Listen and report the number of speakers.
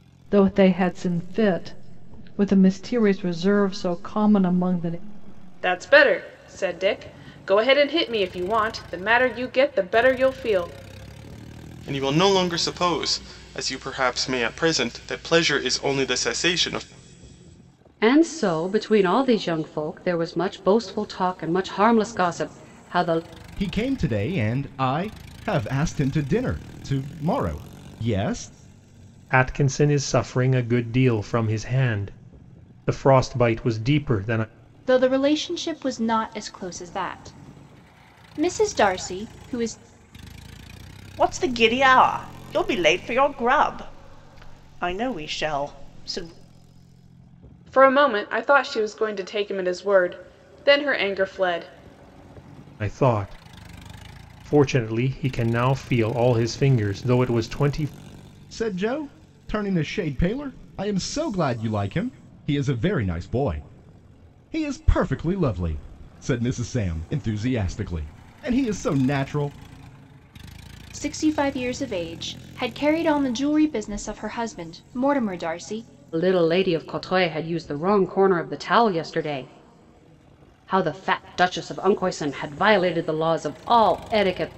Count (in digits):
8